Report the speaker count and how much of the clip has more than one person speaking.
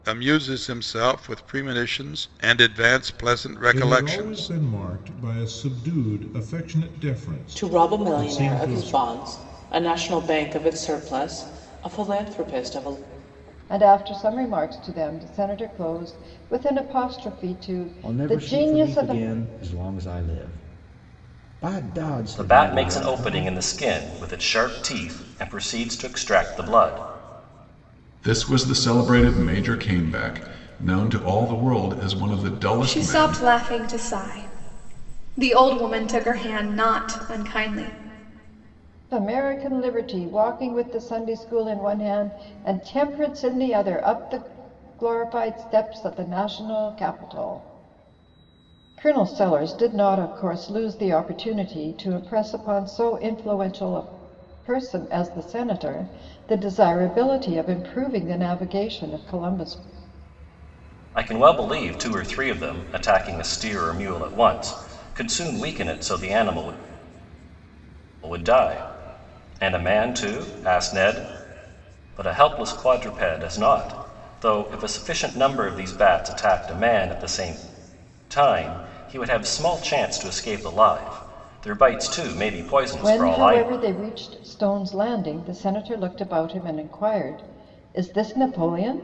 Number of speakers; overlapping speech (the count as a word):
eight, about 7%